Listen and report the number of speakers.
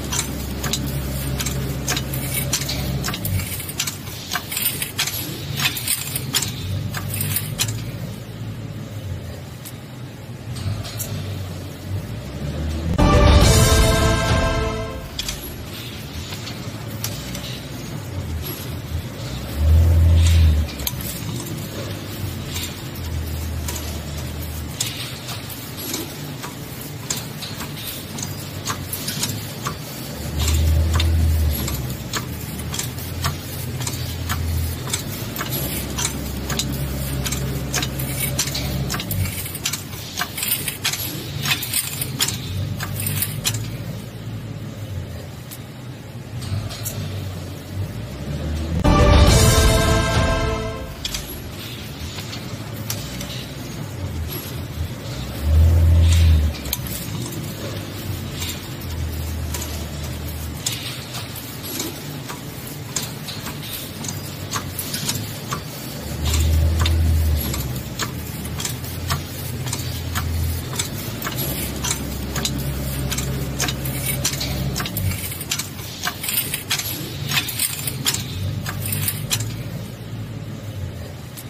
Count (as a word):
zero